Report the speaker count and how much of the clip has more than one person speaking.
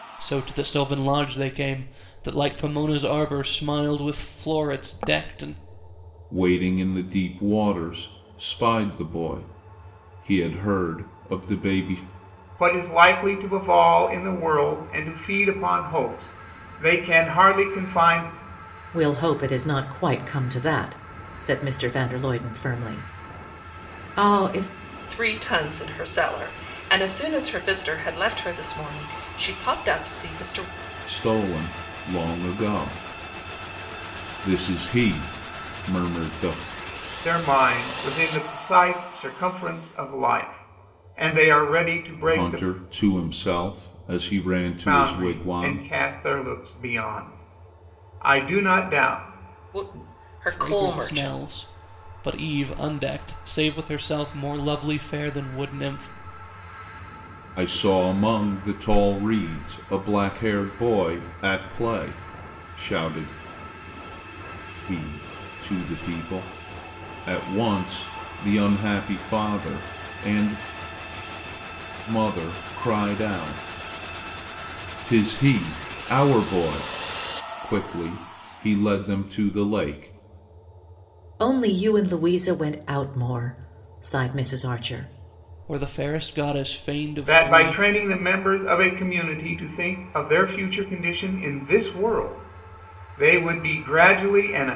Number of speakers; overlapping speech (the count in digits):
5, about 3%